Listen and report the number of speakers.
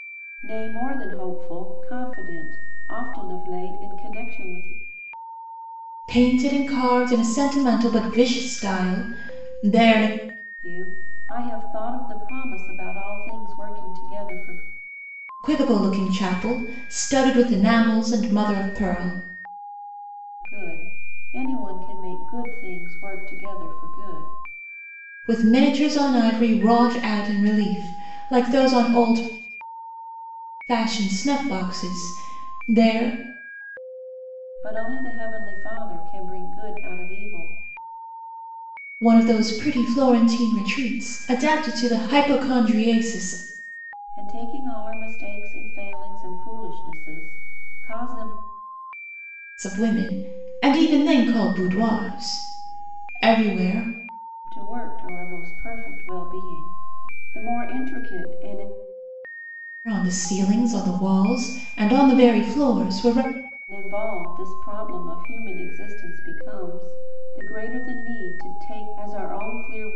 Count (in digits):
2